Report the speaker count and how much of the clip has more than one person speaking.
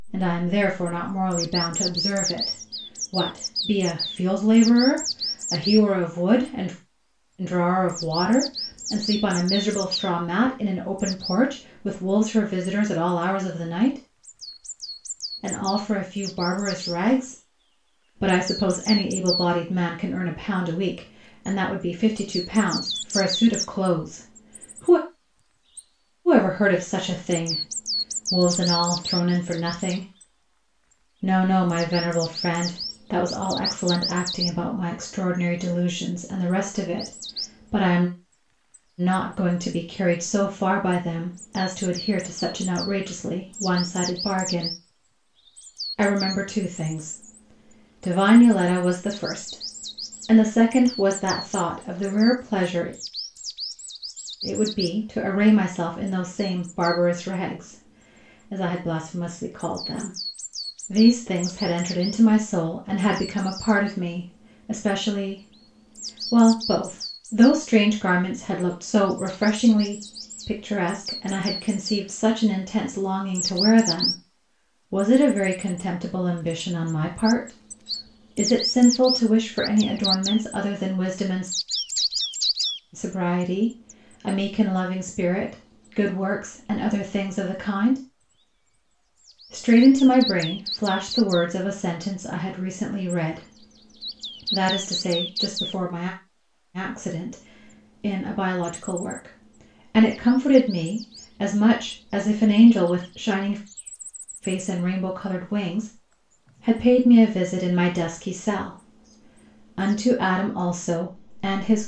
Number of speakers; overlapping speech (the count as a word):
one, no overlap